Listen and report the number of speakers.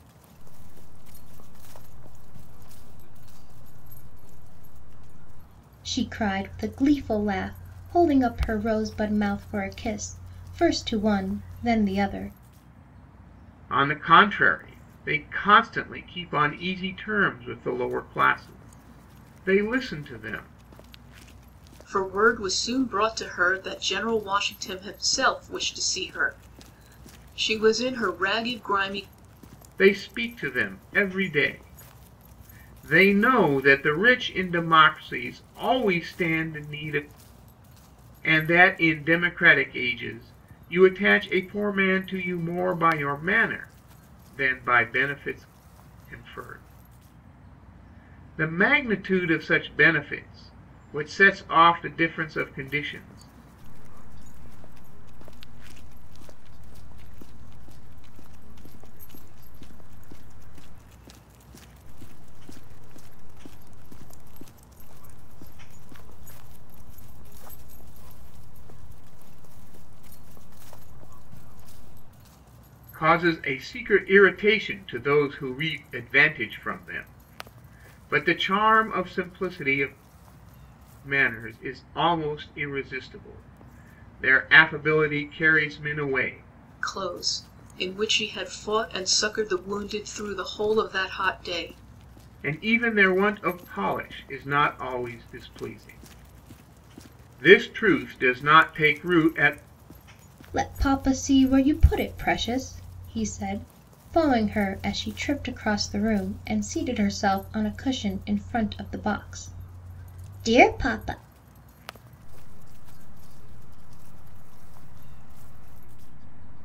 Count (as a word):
four